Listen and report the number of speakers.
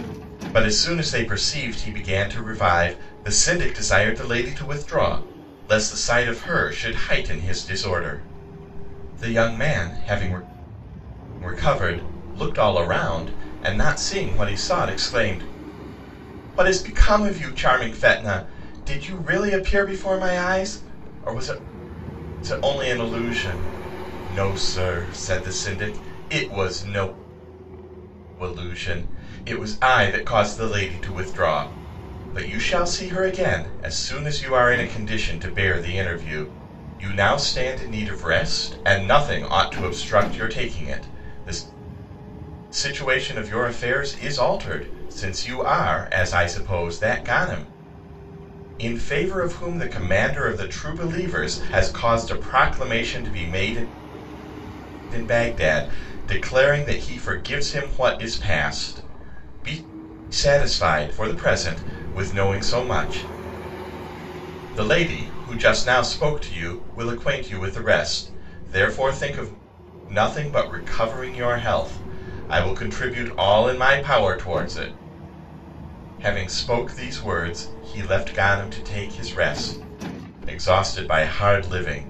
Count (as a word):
one